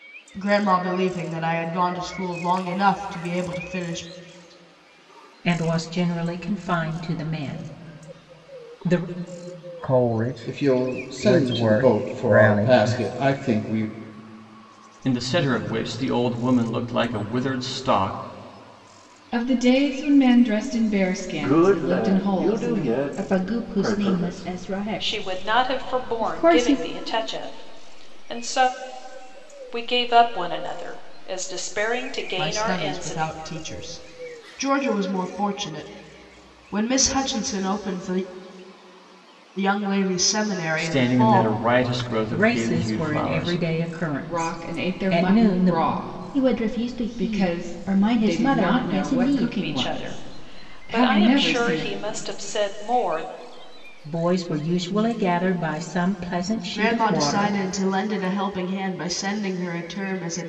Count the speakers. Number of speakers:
nine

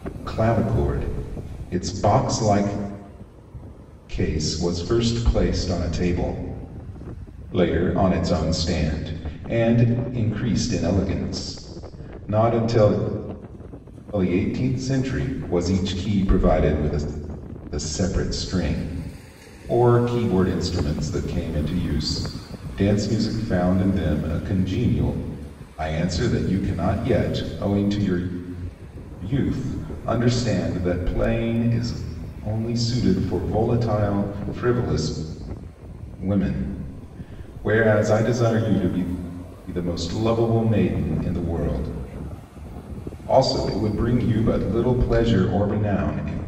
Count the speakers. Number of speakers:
one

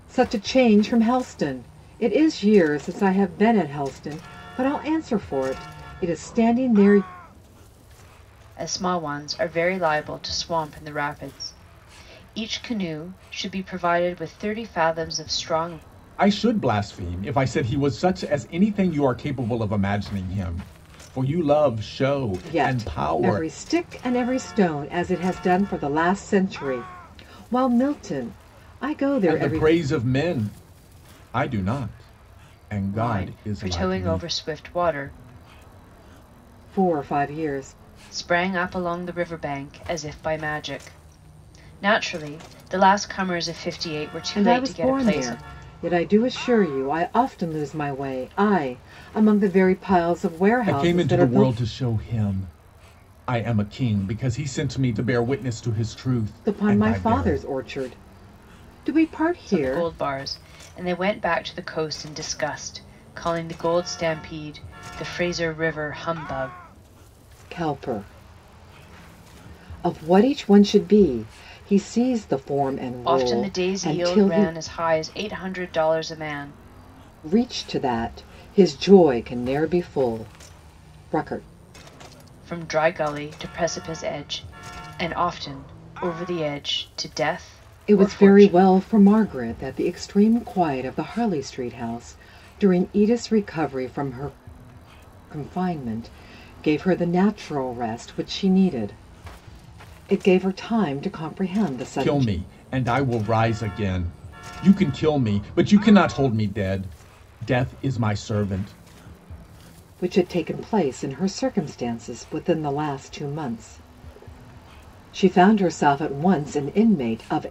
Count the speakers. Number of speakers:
three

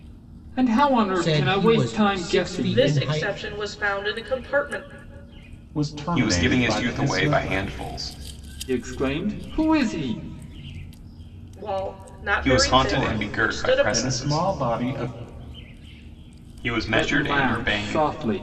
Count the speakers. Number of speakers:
five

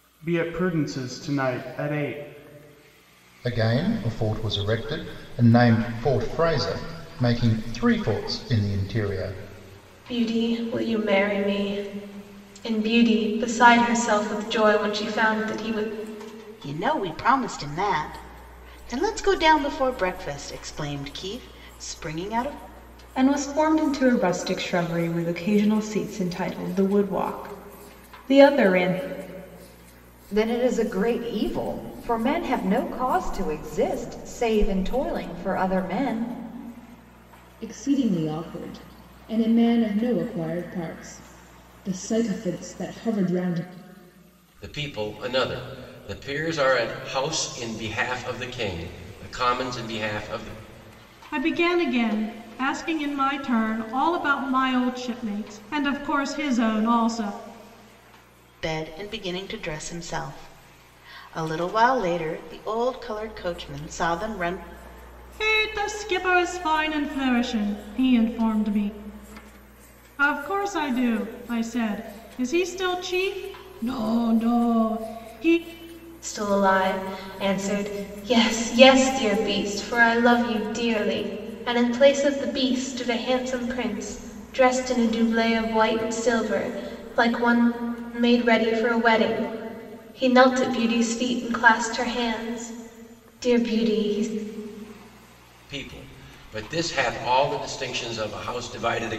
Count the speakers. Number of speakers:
nine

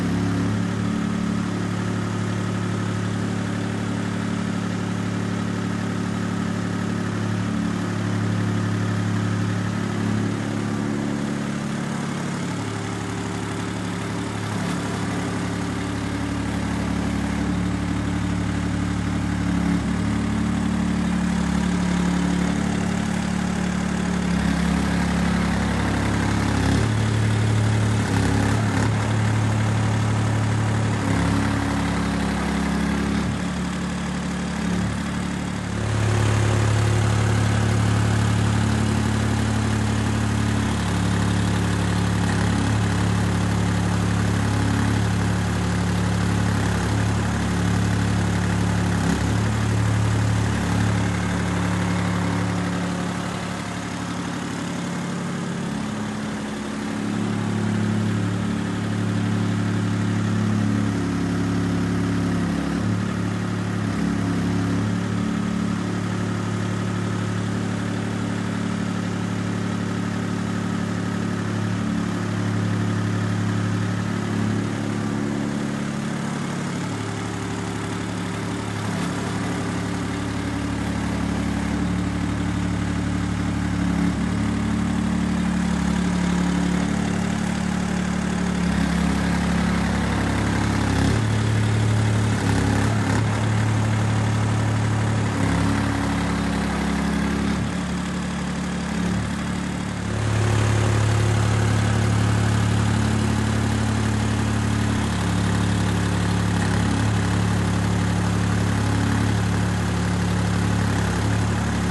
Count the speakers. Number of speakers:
zero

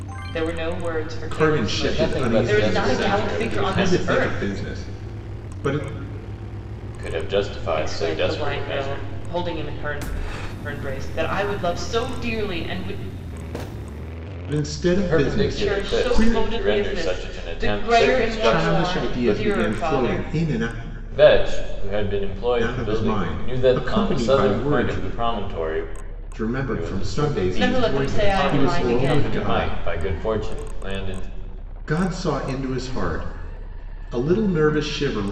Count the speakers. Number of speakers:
three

